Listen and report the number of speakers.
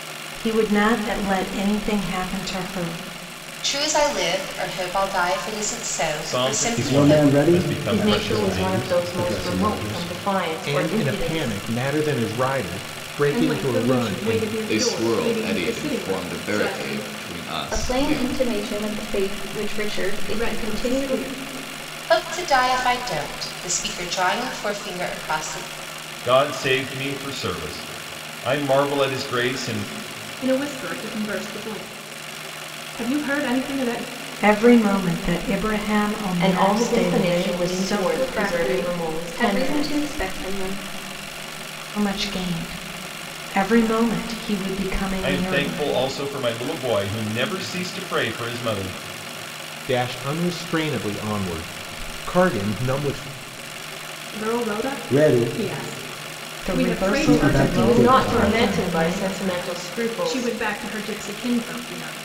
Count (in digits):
9